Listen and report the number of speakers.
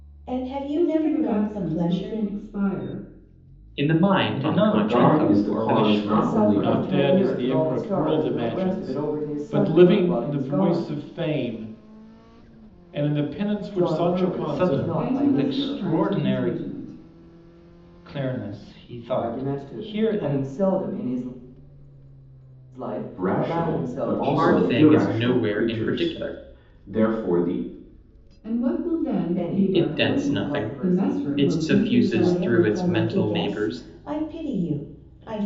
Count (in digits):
7